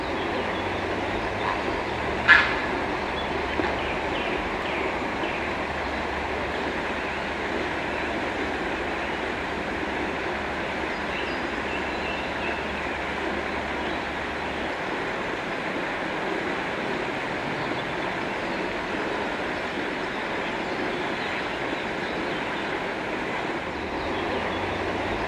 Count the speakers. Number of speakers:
0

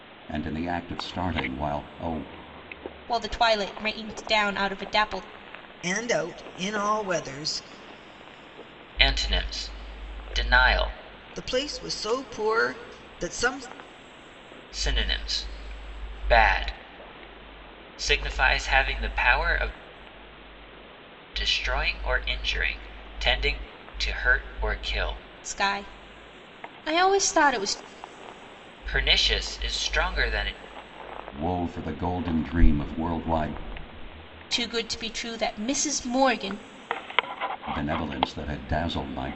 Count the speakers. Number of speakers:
4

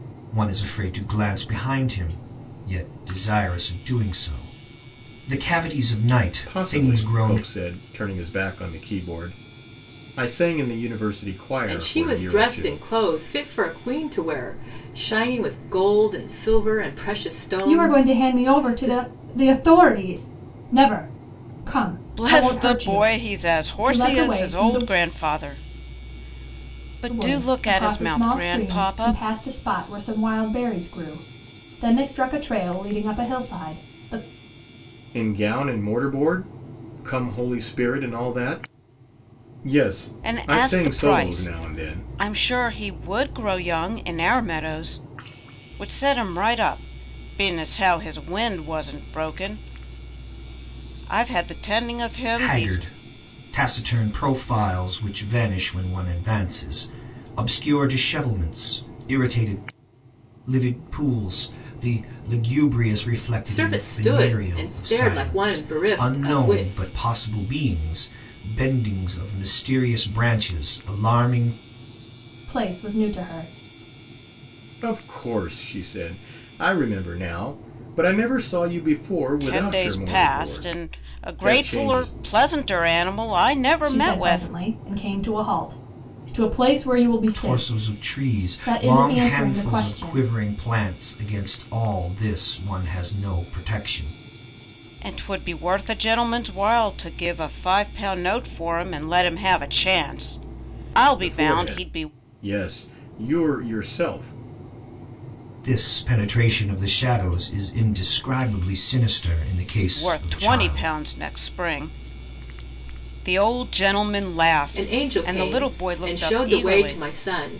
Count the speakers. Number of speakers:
5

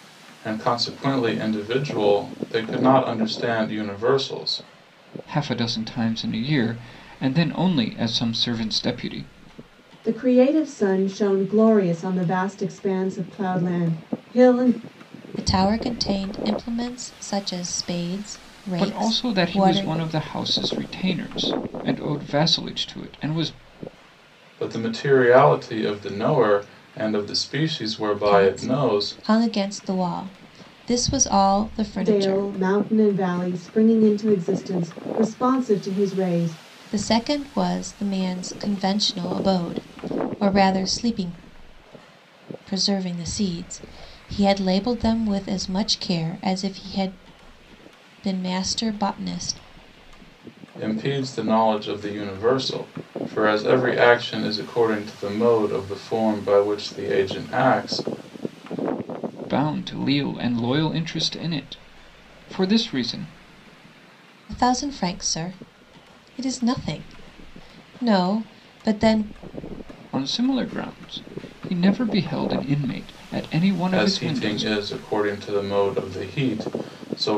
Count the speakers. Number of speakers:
4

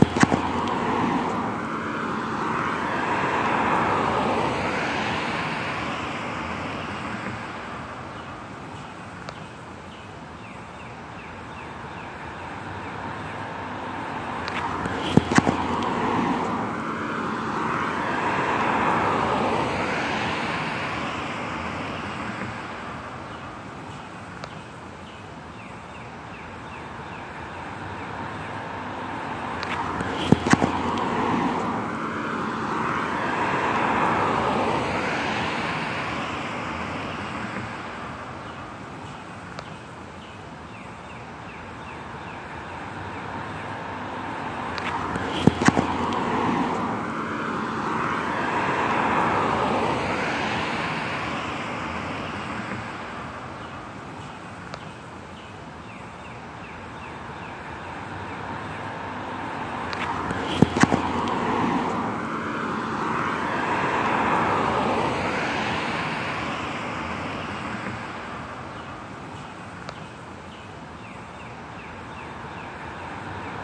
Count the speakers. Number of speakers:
0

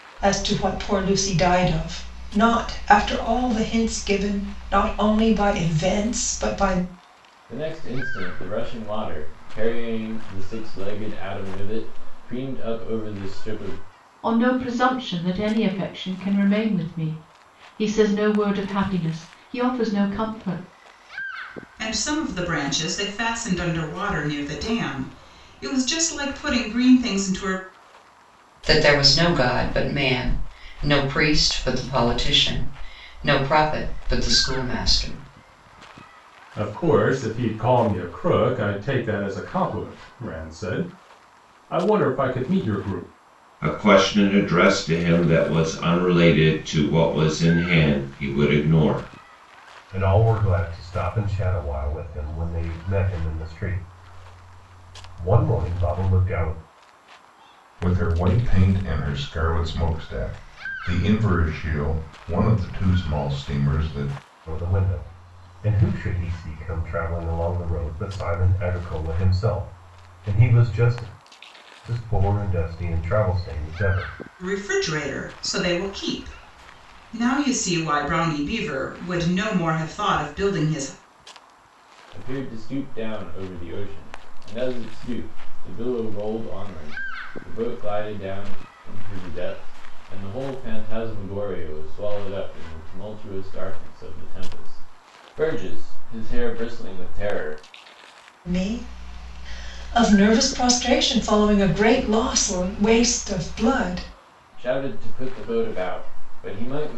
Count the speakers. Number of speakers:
9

